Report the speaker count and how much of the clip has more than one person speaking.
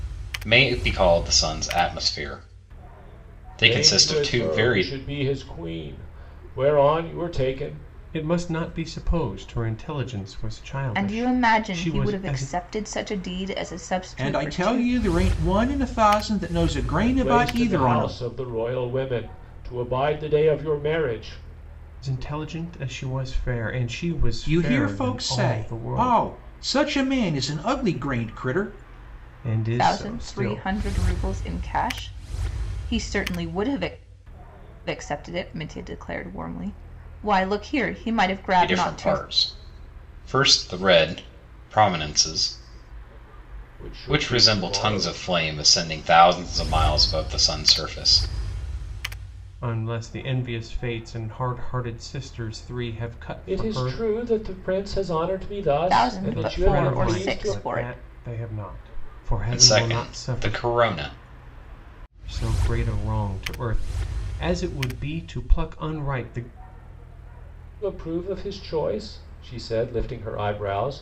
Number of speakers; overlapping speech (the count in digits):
5, about 19%